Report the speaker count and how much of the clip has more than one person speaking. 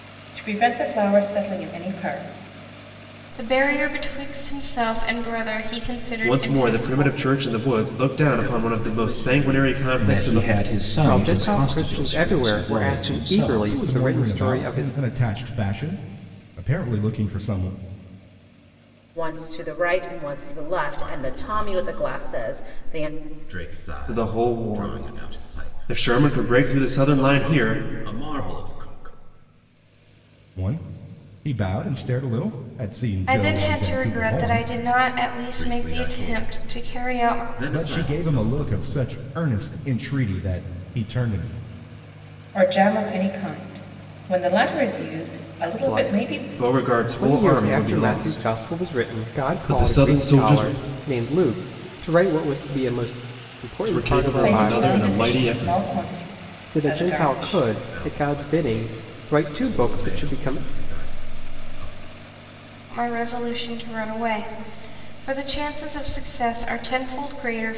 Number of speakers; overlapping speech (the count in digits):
8, about 43%